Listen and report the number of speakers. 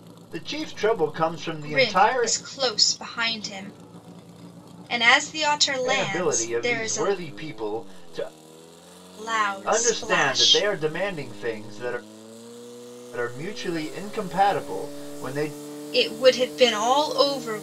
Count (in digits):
2